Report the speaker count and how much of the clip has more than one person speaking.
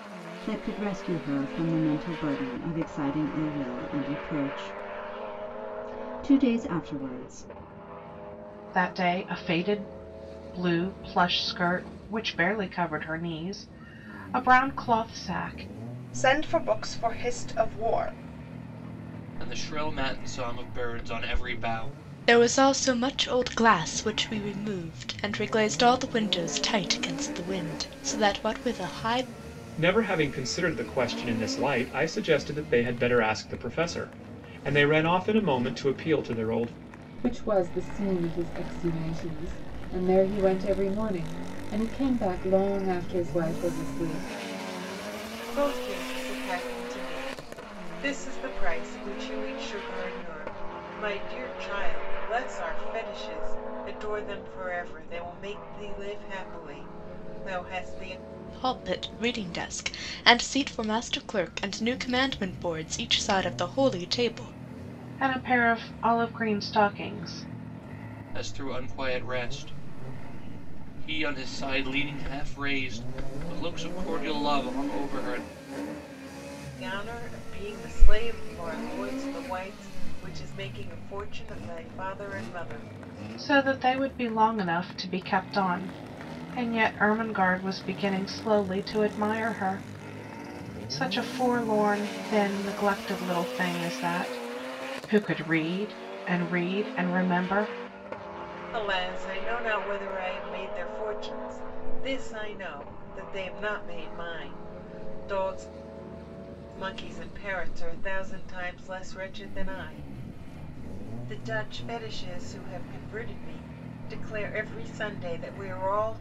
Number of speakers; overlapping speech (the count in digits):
8, no overlap